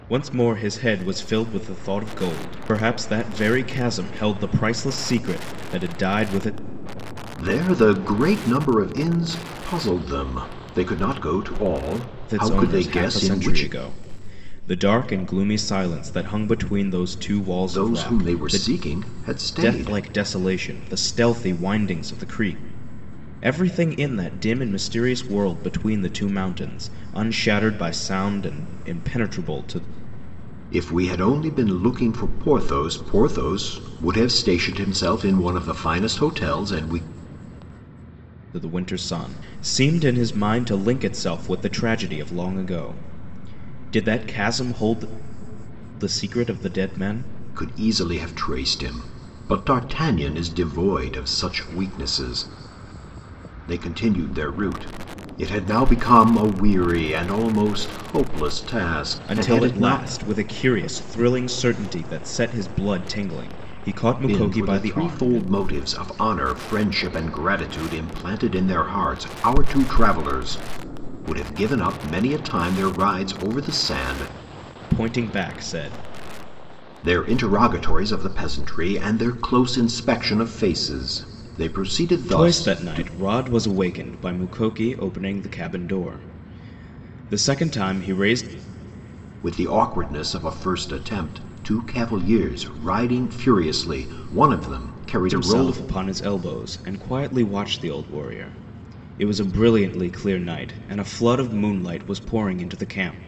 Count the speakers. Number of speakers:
2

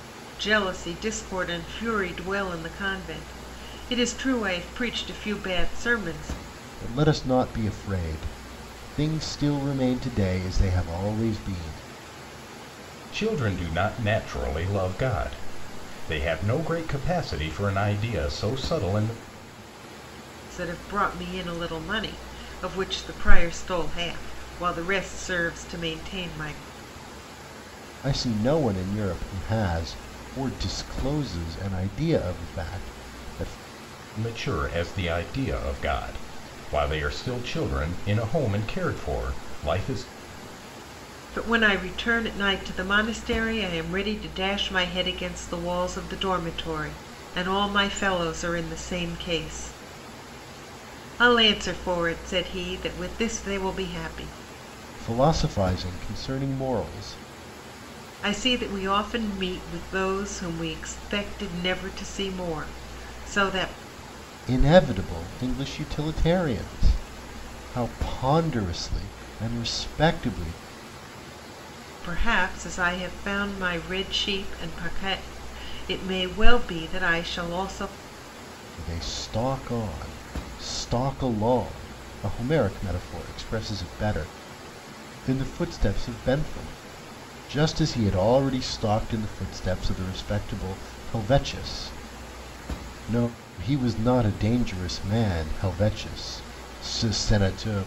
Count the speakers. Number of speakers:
3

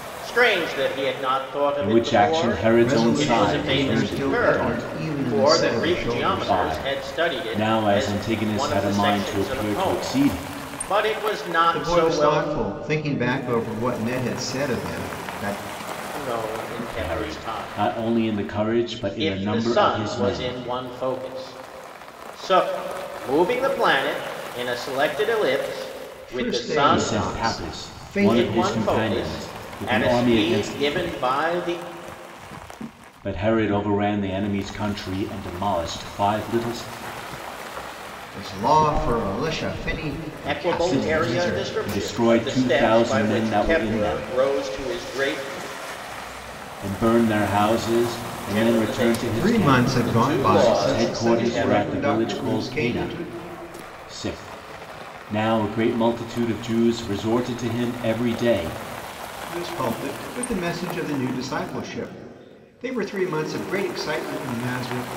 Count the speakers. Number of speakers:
3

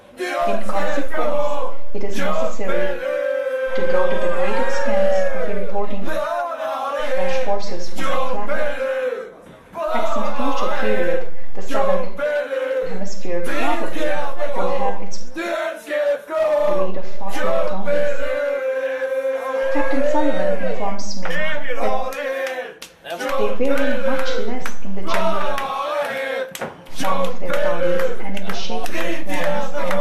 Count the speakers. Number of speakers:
1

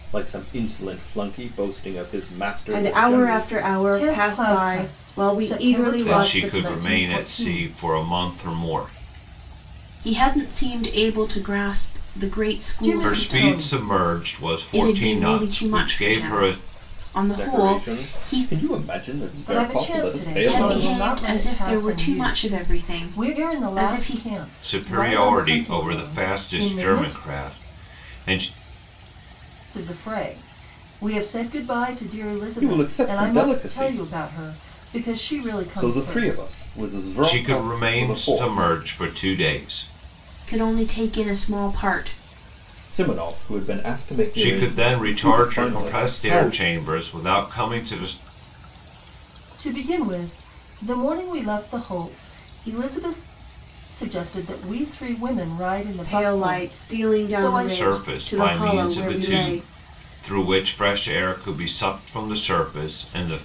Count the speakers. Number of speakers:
5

